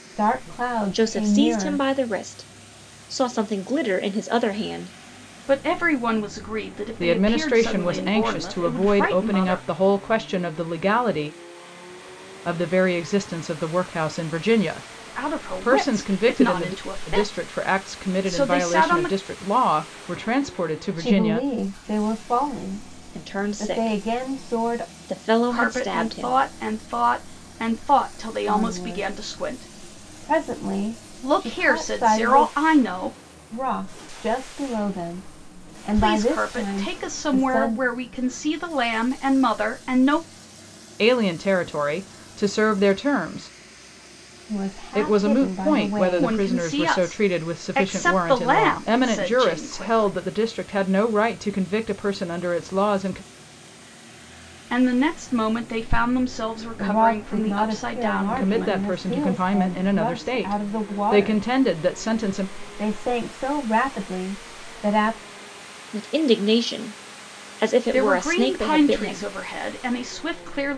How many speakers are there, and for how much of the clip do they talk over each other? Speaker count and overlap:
4, about 39%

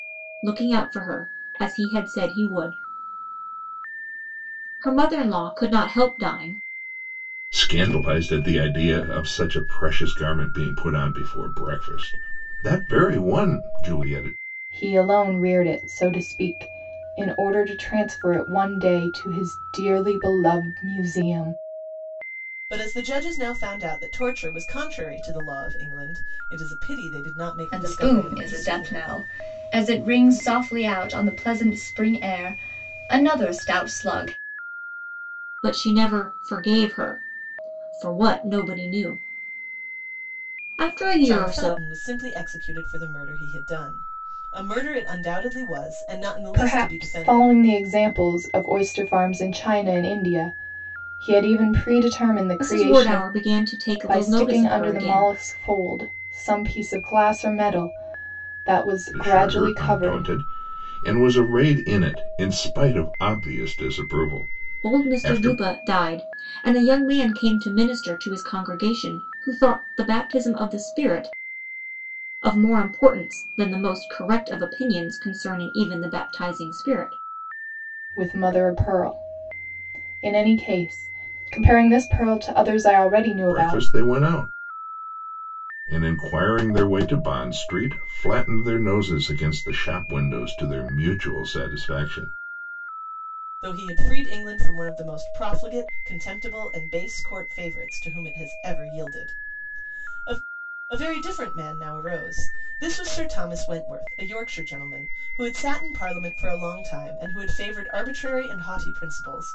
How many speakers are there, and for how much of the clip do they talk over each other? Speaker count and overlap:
5, about 7%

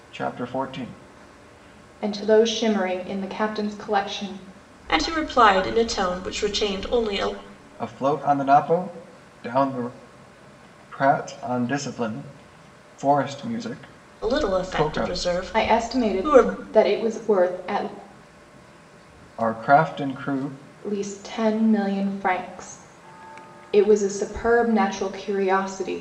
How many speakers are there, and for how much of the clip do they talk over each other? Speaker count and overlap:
3, about 7%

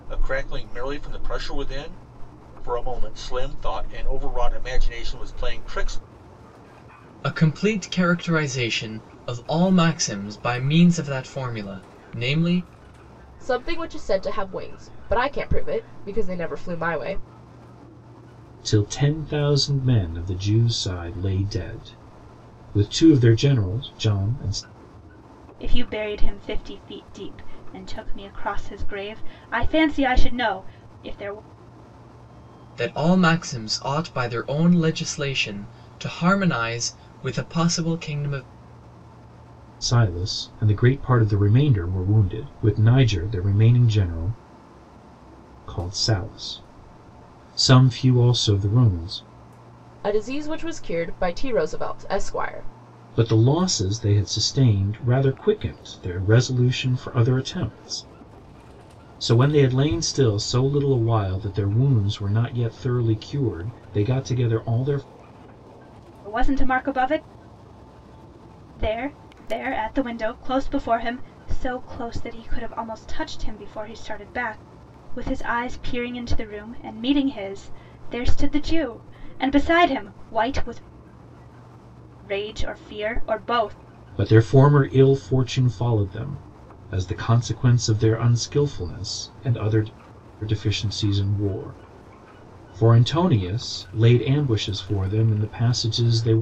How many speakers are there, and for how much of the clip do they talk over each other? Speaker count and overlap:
5, no overlap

